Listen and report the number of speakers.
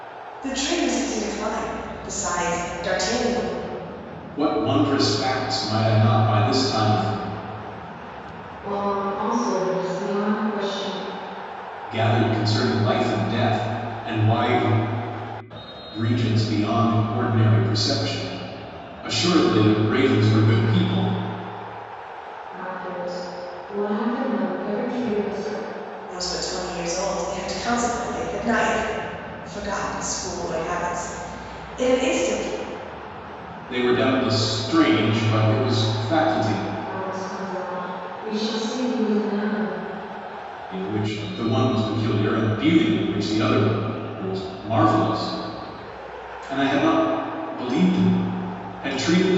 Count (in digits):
3